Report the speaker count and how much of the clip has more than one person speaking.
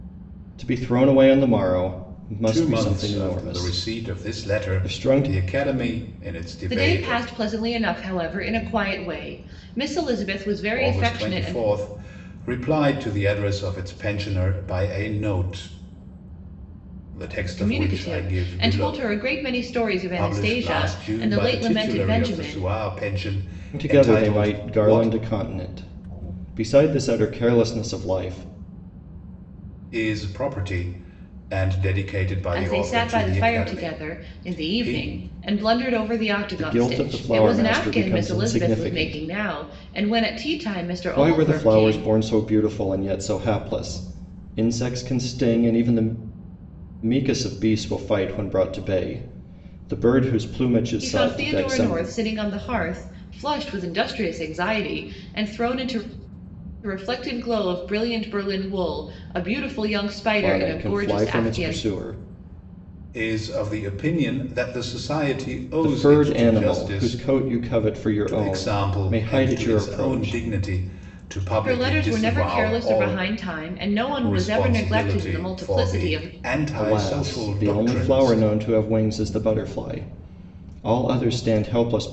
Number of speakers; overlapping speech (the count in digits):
3, about 34%